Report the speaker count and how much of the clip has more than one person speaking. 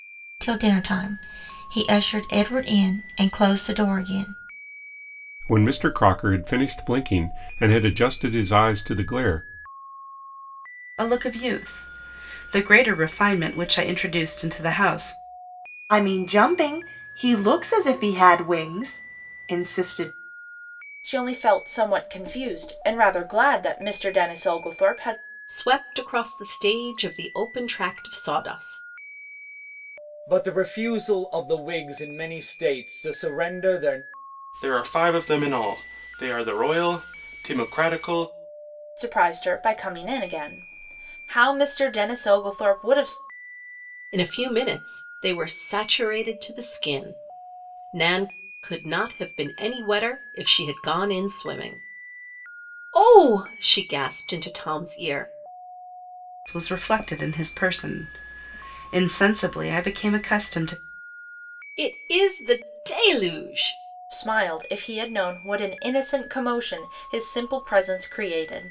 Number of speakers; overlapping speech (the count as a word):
eight, no overlap